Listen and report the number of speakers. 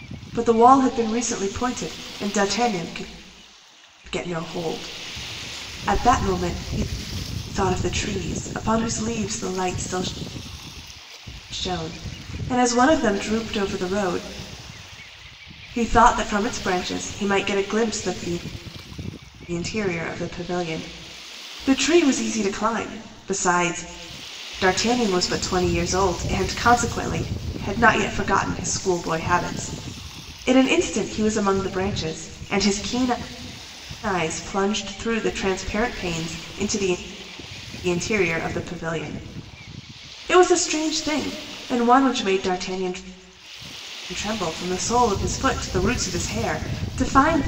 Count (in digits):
1